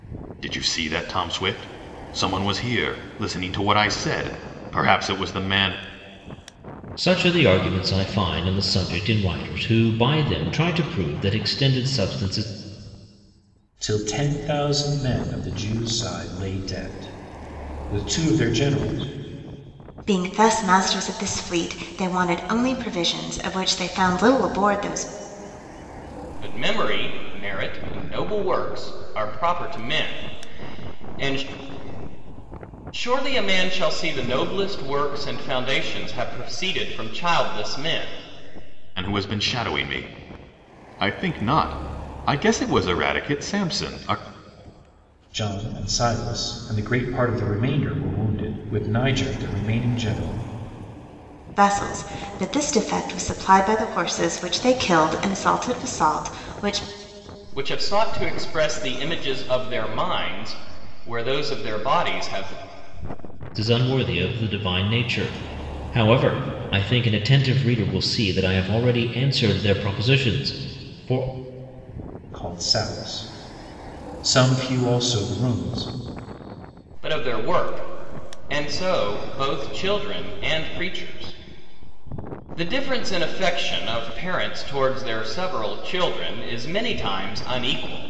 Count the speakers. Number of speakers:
five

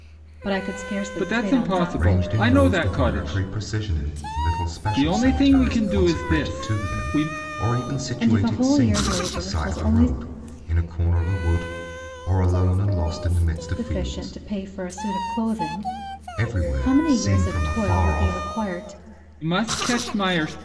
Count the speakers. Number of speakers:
three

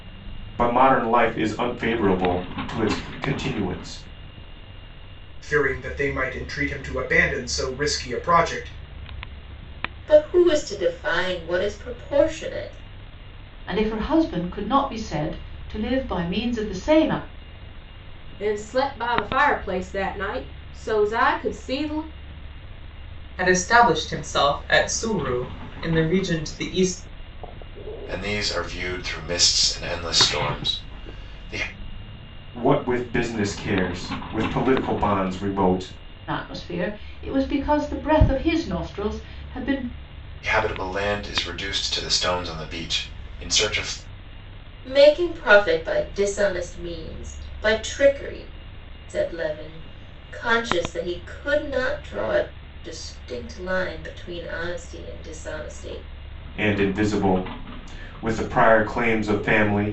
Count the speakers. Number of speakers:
seven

